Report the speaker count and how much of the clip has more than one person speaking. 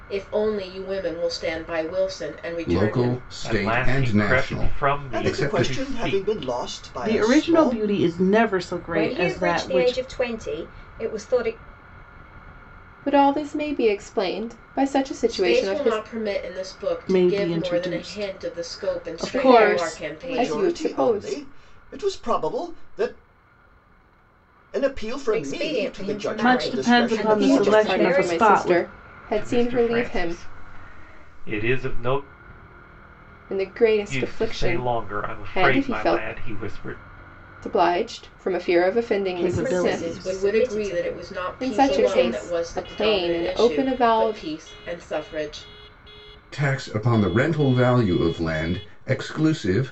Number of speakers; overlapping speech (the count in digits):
7, about 46%